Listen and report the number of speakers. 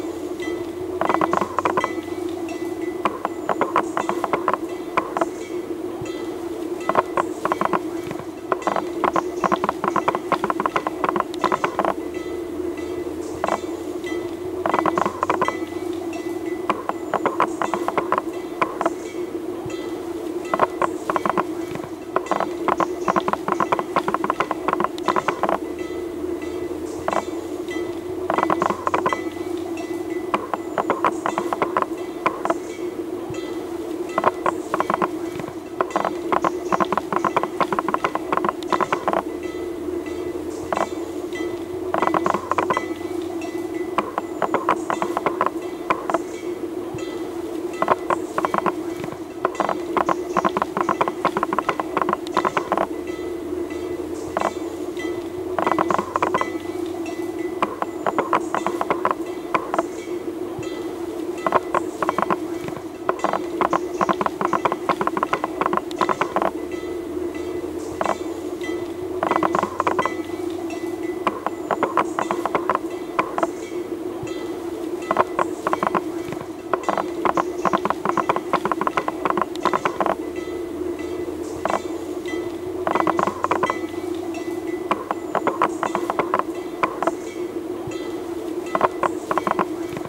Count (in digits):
0